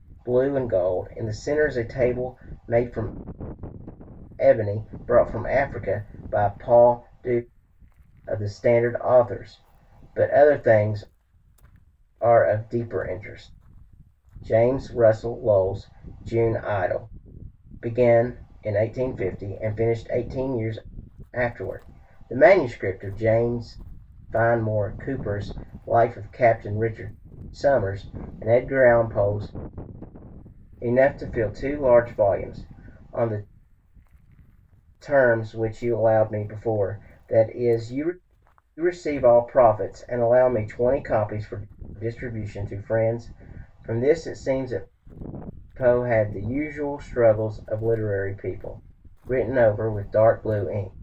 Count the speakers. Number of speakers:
one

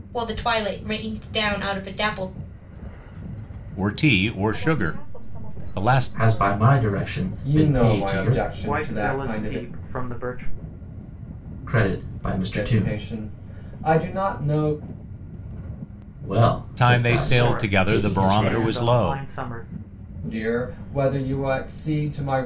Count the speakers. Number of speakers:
six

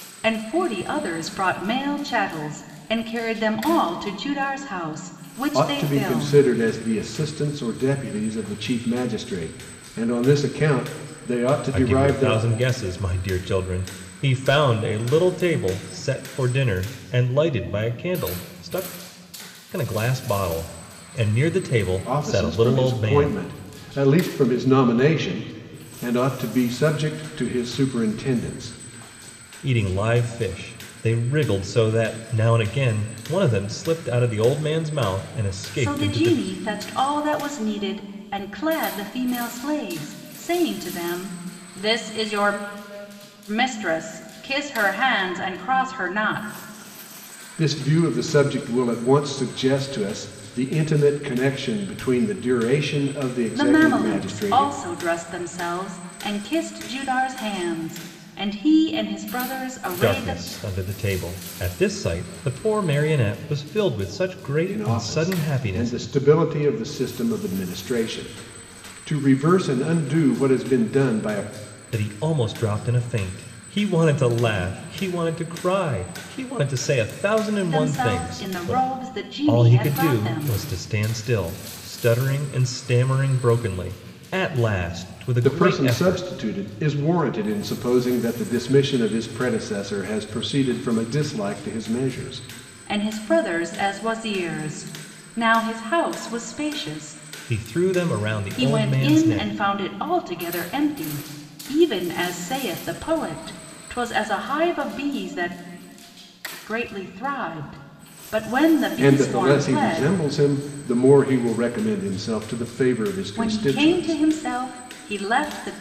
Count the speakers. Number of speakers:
three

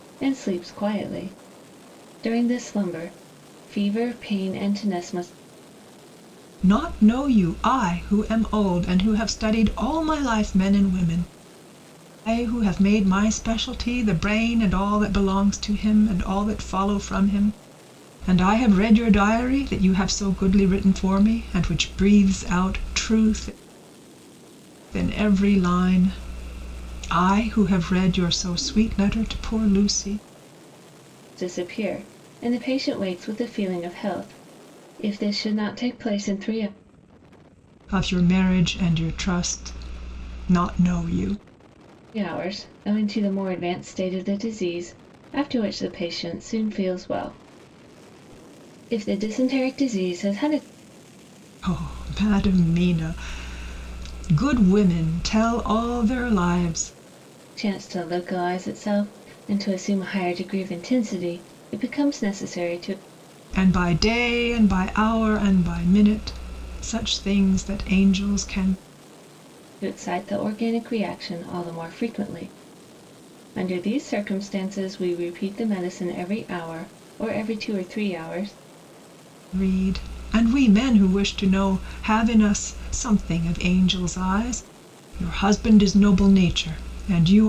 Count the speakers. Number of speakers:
two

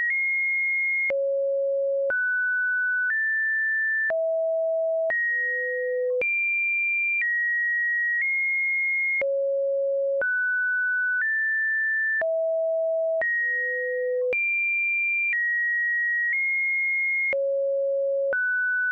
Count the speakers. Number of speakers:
zero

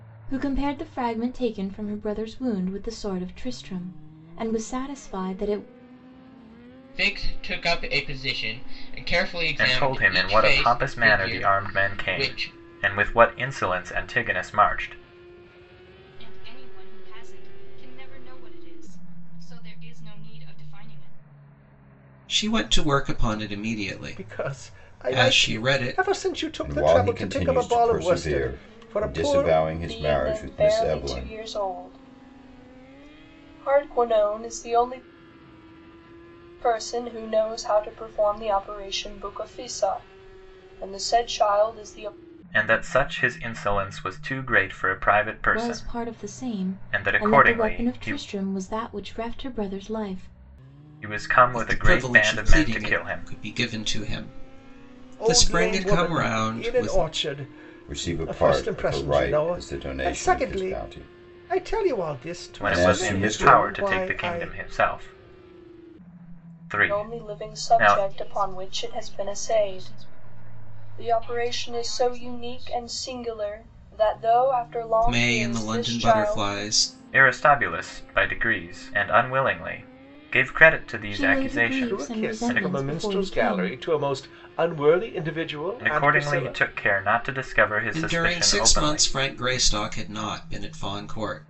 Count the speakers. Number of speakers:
eight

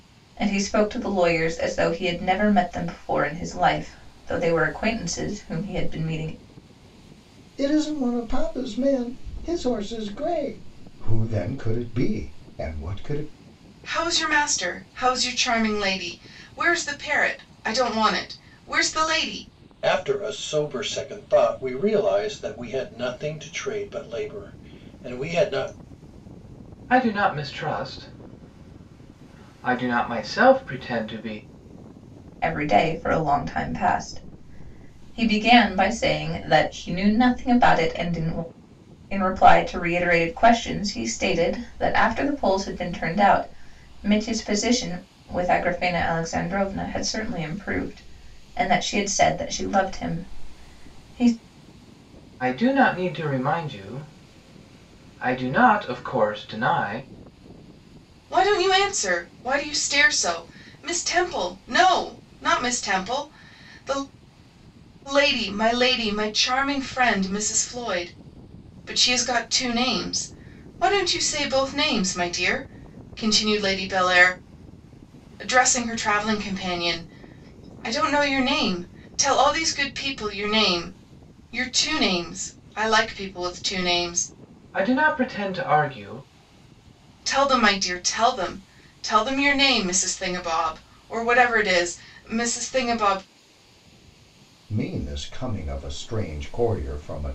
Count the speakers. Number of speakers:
five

